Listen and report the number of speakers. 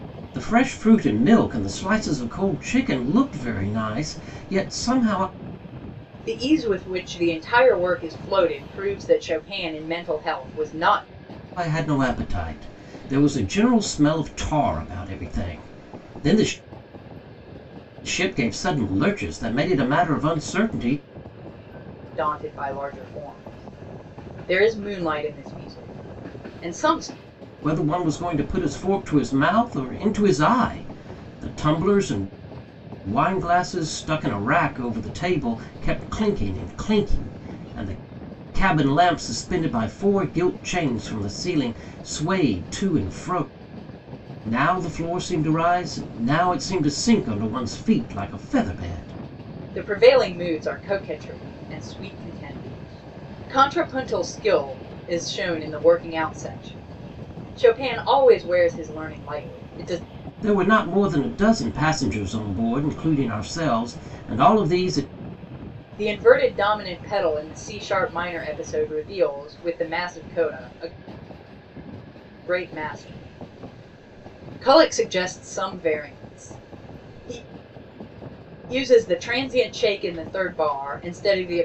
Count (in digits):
2